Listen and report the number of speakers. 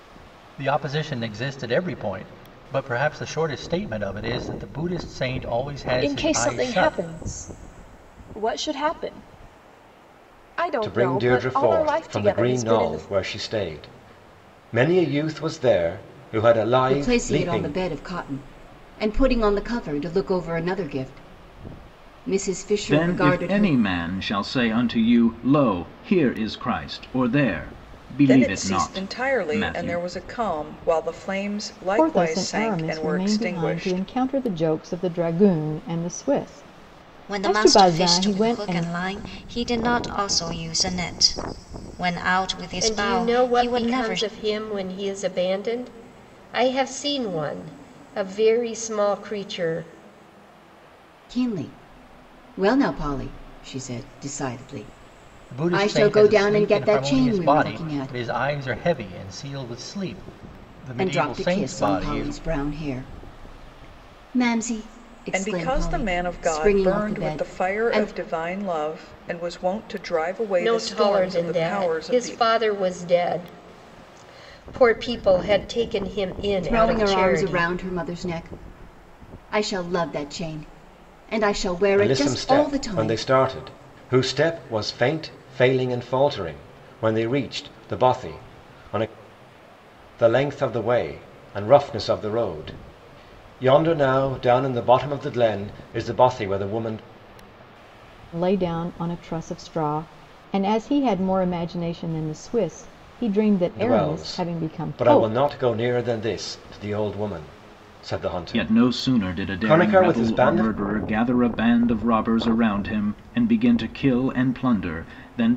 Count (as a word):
nine